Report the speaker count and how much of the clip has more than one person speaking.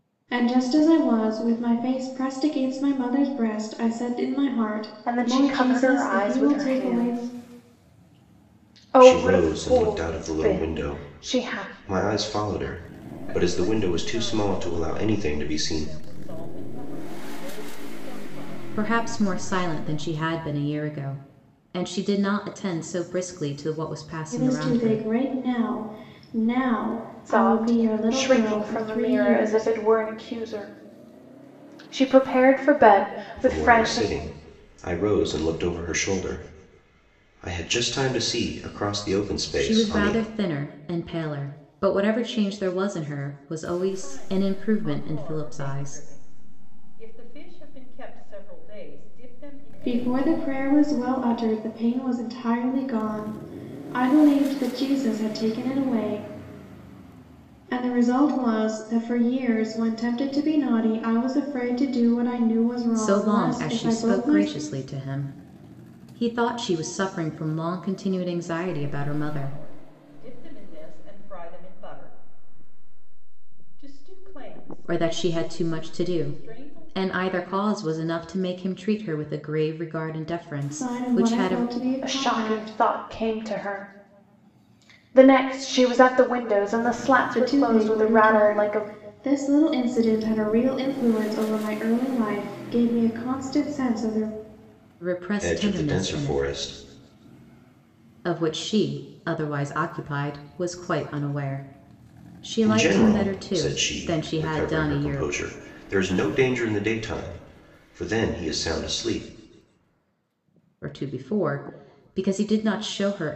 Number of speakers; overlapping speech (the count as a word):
five, about 25%